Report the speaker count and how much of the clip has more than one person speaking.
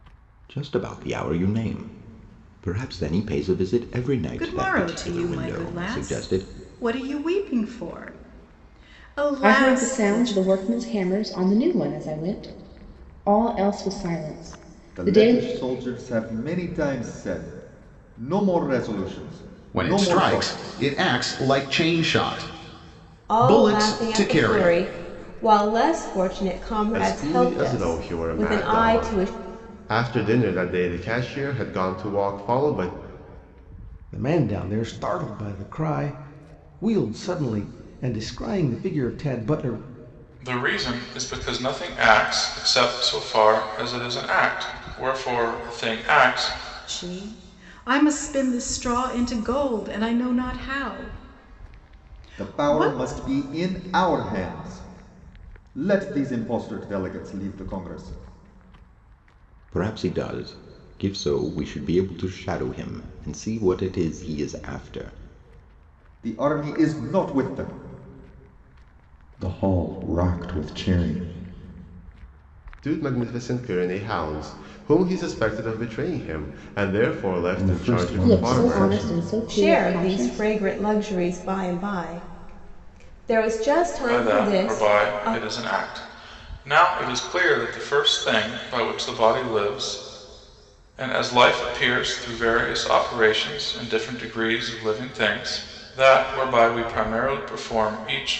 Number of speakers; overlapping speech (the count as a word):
nine, about 14%